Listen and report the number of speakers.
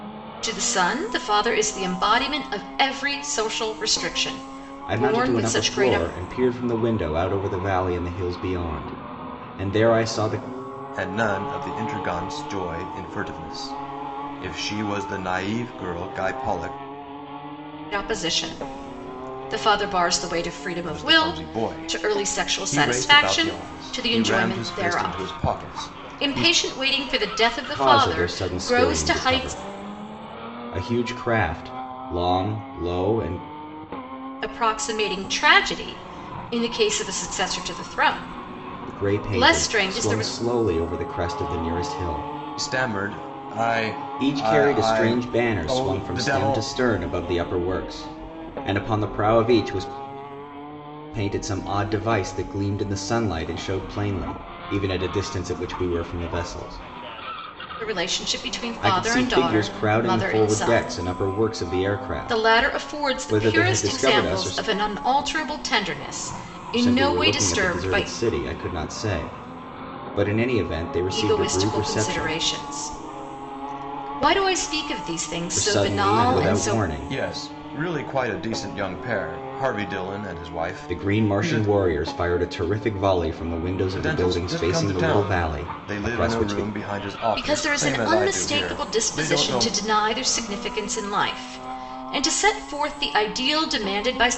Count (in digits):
3